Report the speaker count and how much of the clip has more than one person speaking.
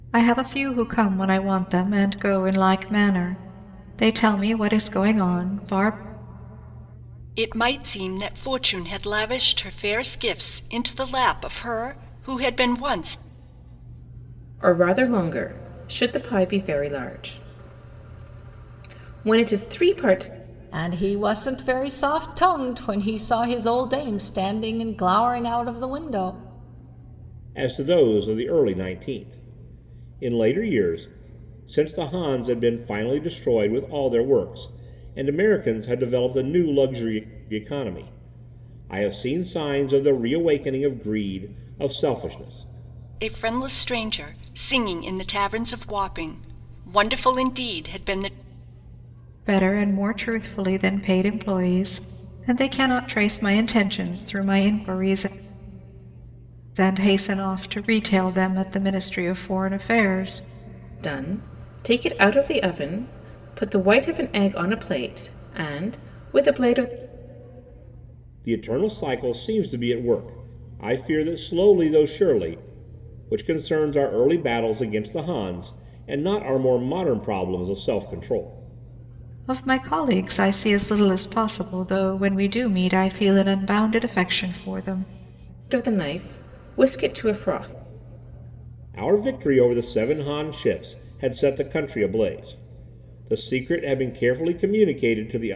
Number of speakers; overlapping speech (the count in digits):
5, no overlap